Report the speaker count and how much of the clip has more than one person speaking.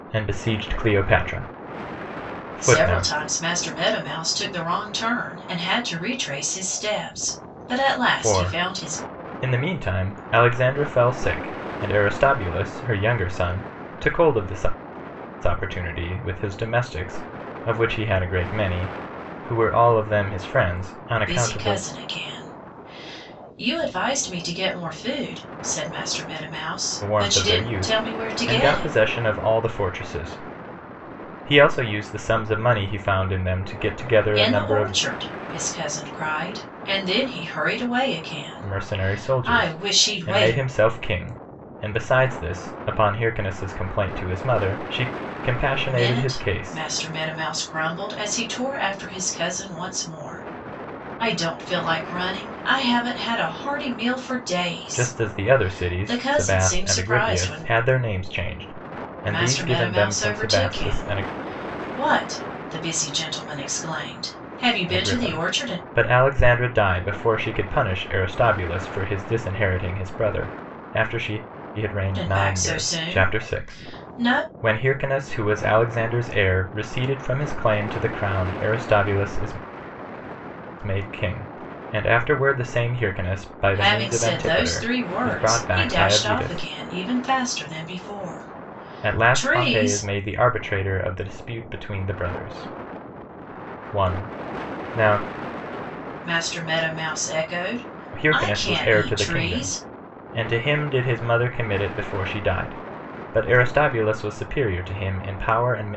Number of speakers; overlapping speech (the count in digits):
2, about 20%